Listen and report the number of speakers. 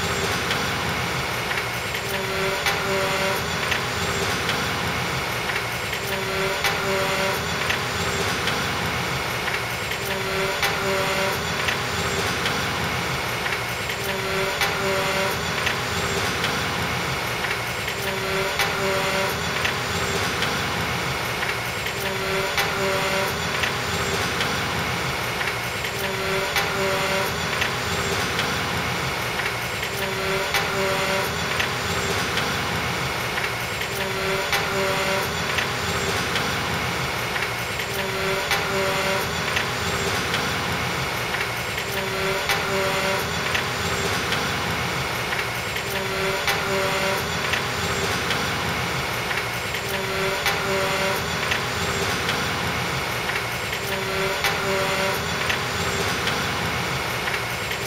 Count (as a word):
zero